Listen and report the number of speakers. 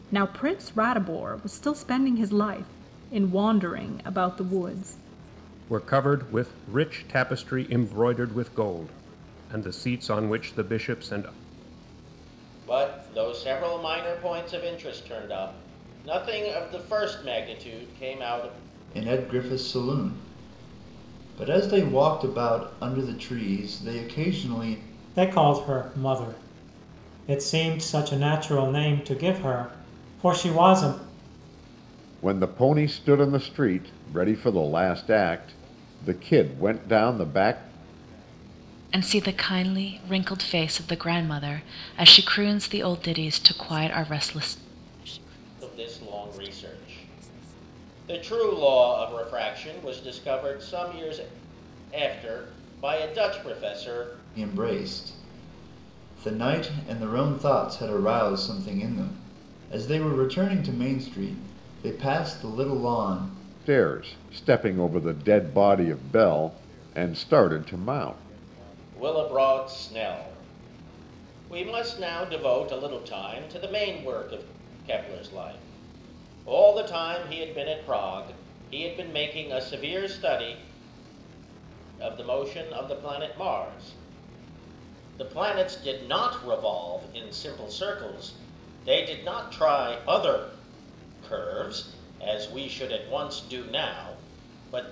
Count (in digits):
7